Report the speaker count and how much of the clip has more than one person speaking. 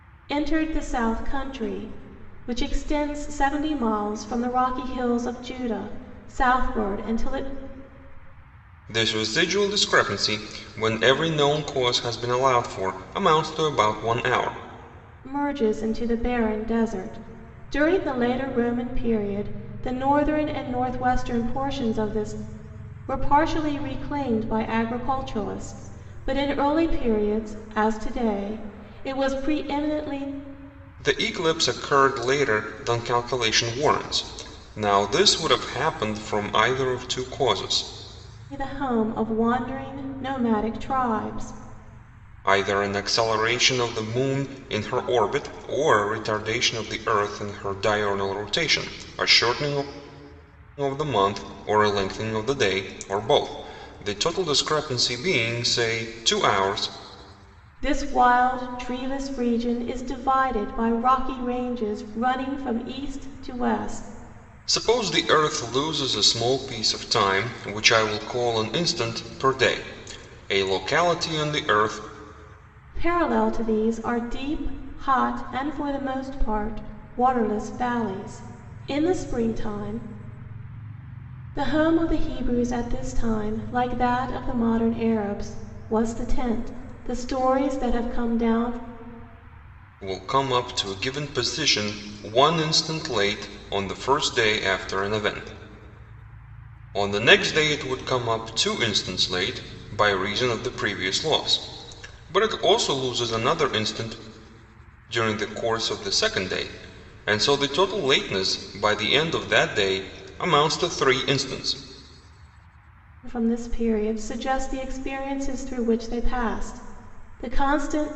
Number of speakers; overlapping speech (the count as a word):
two, no overlap